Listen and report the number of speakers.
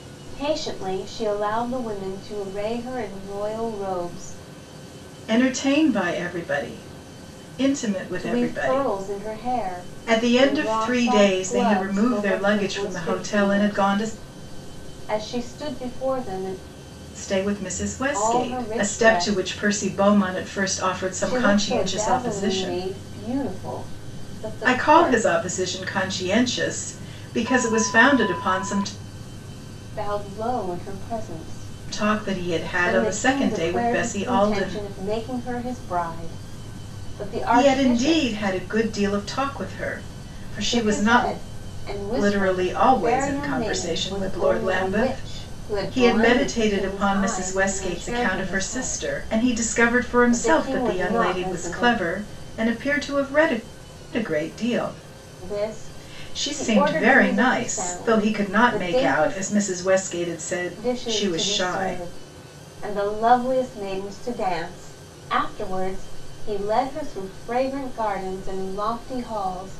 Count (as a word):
two